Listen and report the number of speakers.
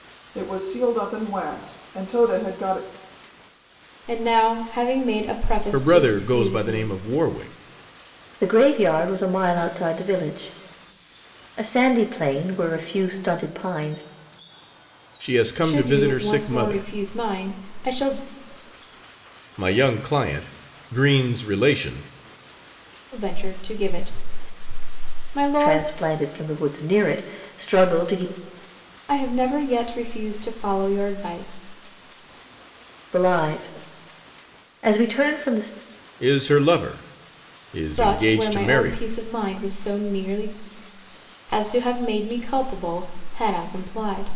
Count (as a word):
four